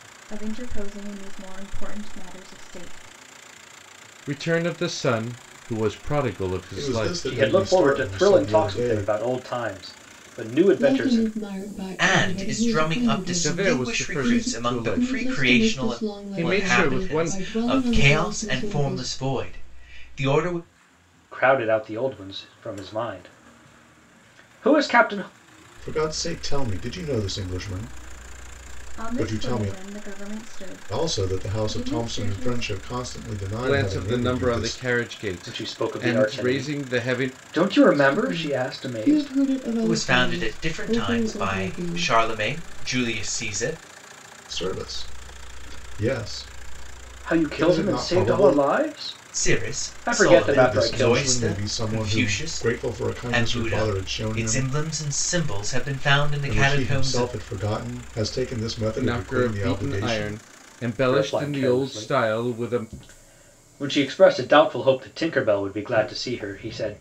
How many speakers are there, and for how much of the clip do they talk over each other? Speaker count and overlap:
6, about 45%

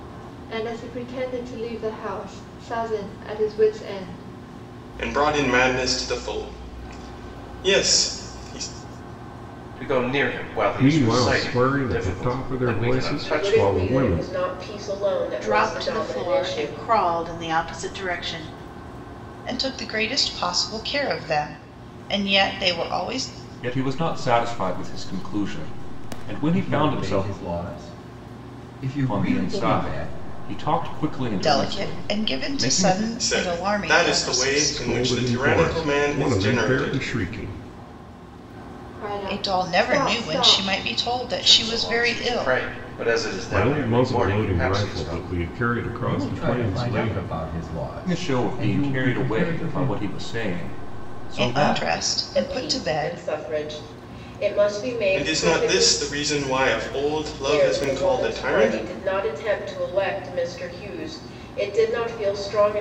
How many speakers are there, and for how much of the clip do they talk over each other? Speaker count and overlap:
9, about 38%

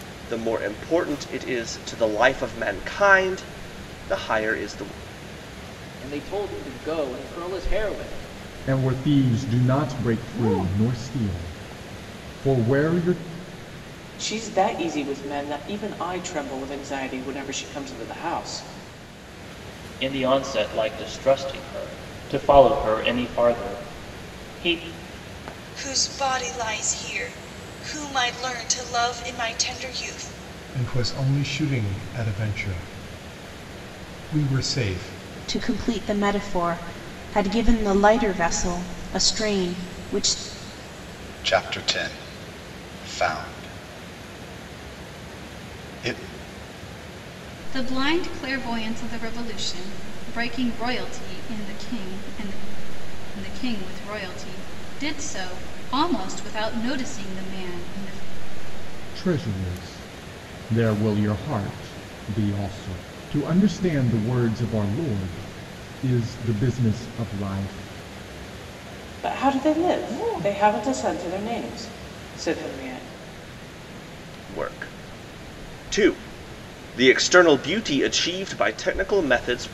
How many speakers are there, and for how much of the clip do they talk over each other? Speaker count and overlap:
10, no overlap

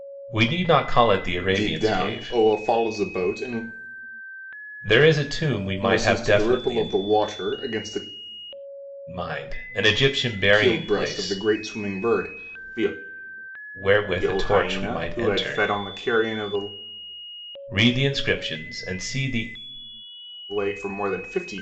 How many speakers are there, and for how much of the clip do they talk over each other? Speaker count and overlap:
2, about 20%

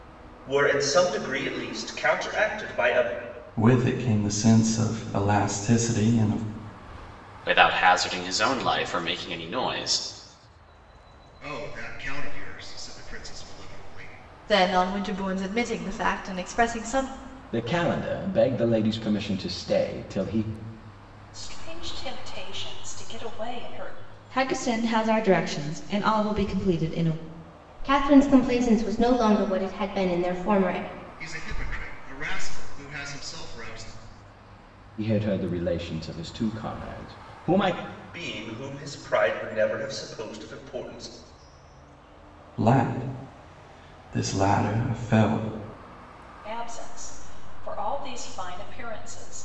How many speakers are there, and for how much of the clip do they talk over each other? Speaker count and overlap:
9, no overlap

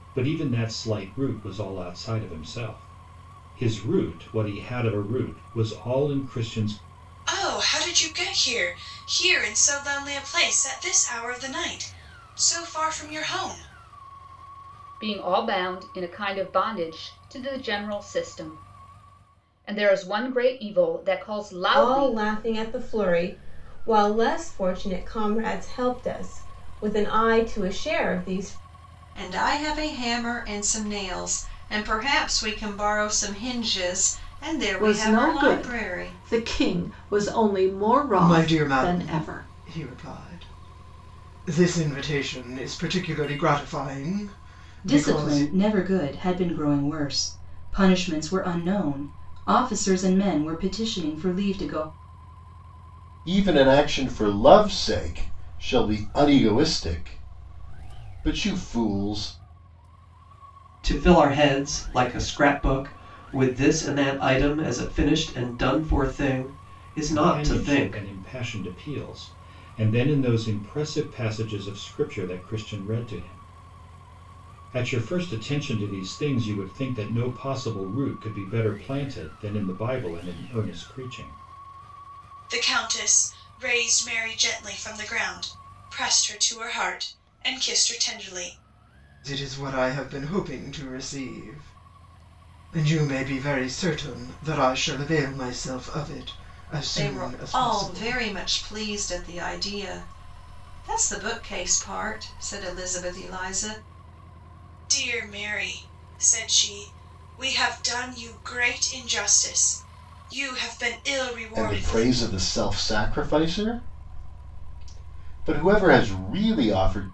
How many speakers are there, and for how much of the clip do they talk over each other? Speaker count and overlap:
10, about 6%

